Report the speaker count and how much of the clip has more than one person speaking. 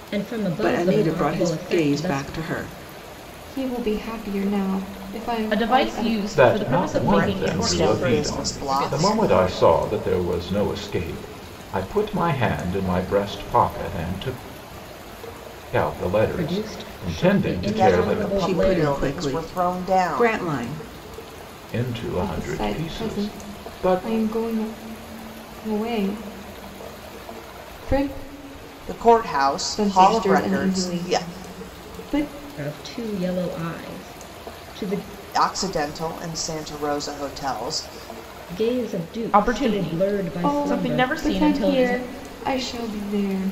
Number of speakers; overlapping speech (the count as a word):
six, about 36%